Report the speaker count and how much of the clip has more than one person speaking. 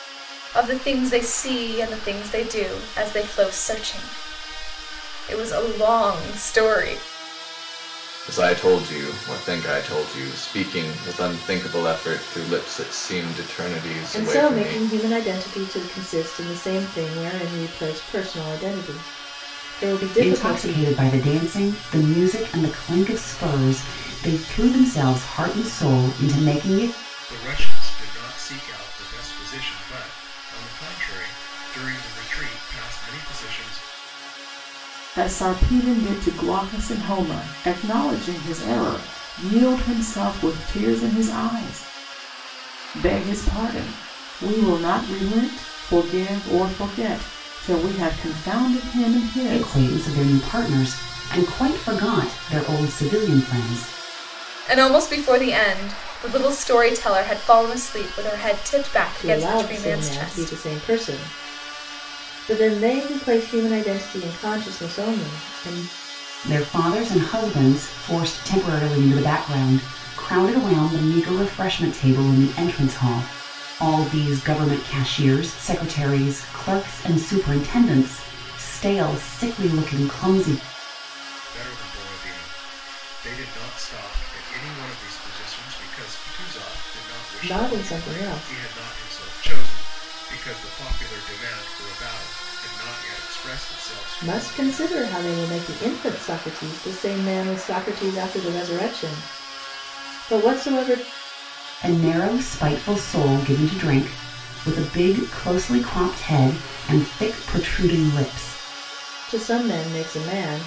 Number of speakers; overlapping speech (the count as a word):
six, about 5%